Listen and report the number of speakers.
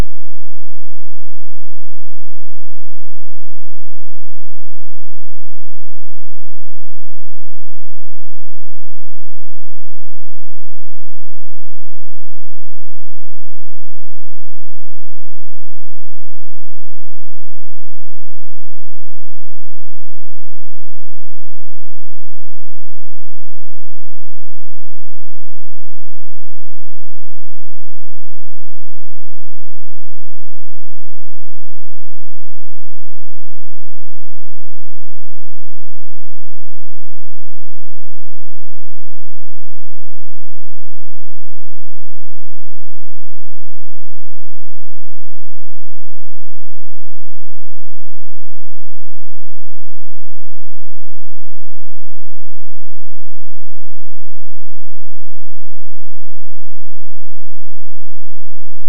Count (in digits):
0